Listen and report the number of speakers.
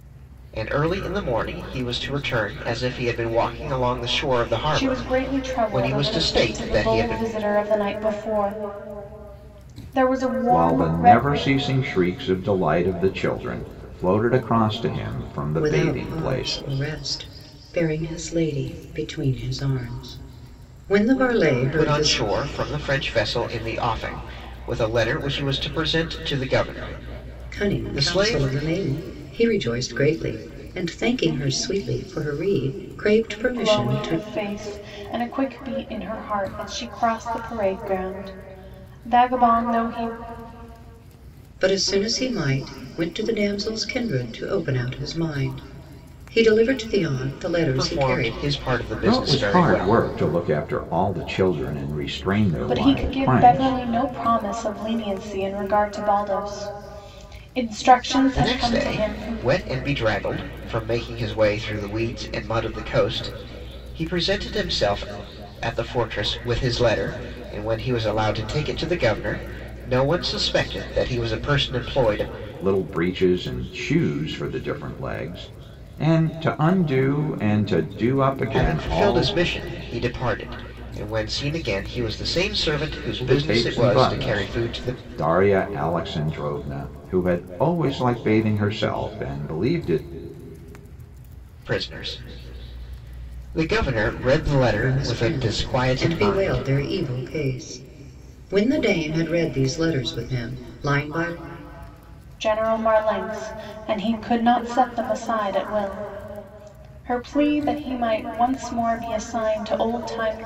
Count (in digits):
4